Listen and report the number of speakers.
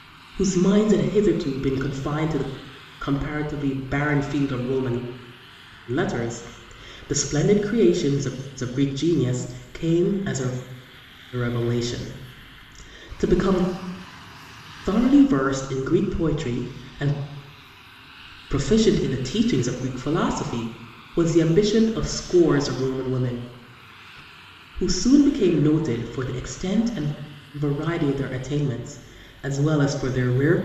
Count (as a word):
one